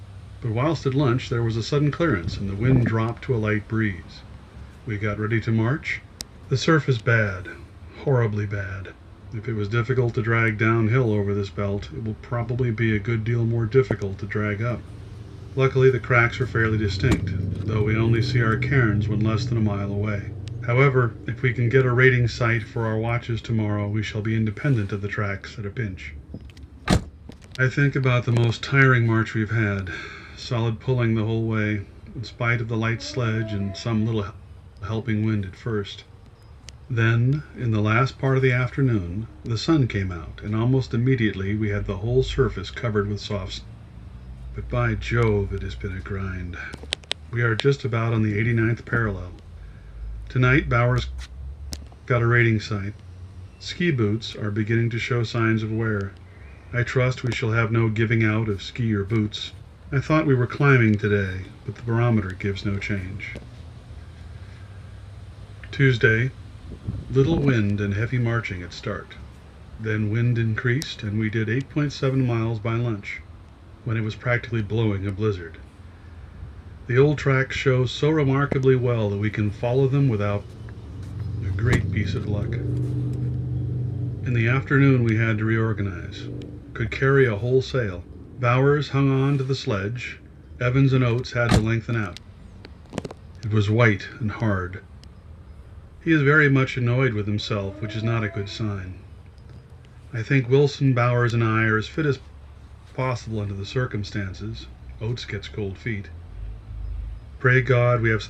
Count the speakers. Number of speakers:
1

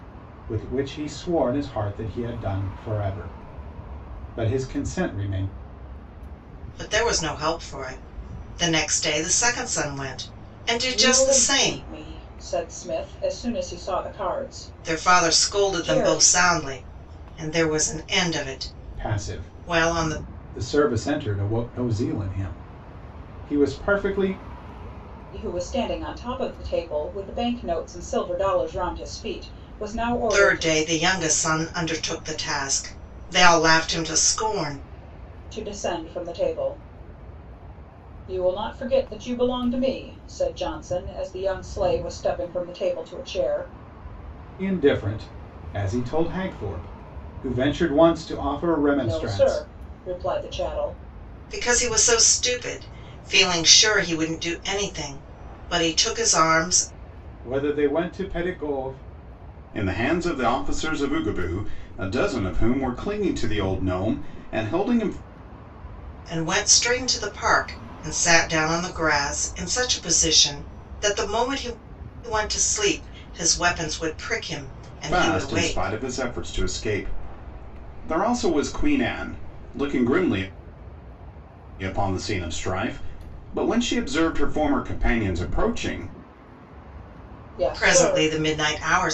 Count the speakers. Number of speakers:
3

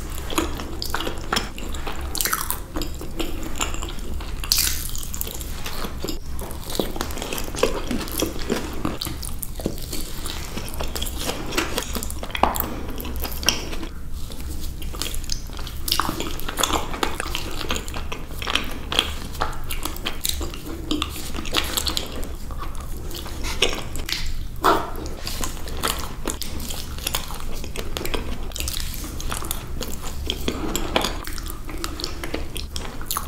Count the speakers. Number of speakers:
0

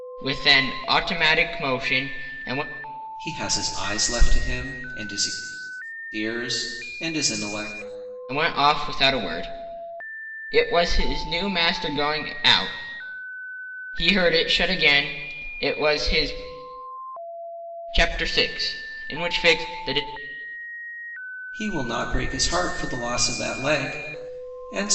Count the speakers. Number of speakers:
2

